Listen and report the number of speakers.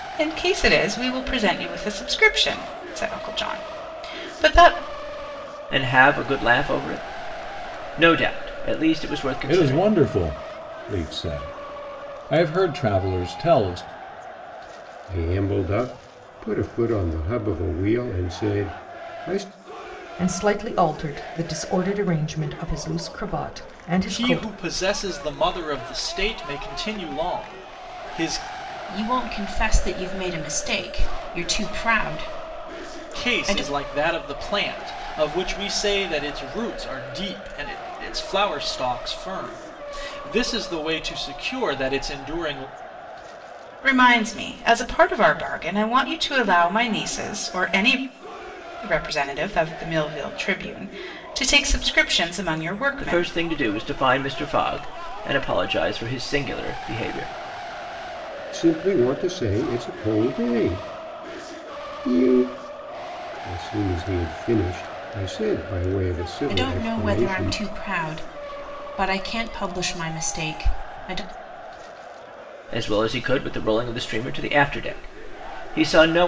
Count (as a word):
seven